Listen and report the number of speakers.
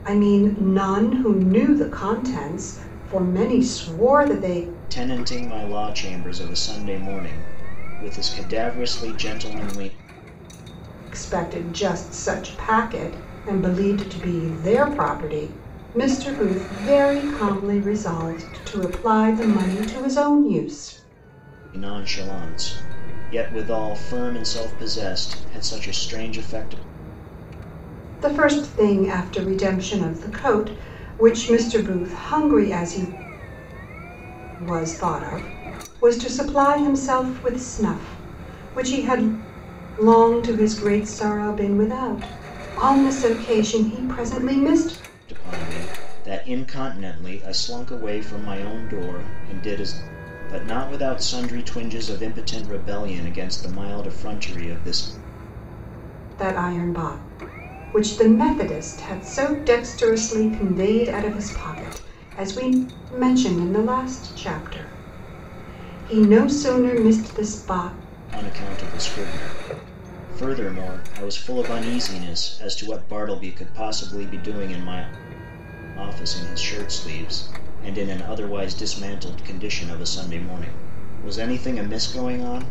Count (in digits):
2